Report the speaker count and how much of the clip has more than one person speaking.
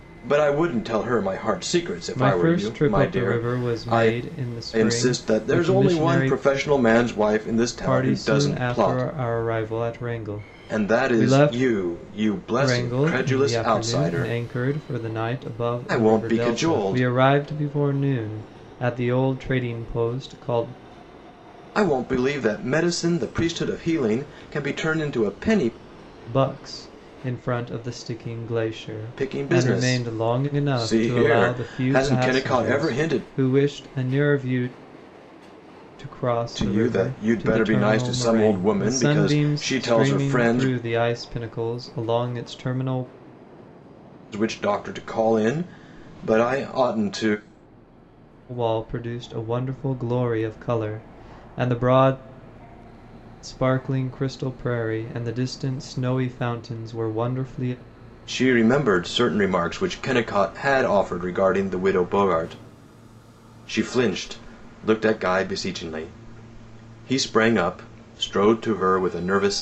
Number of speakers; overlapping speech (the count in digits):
2, about 25%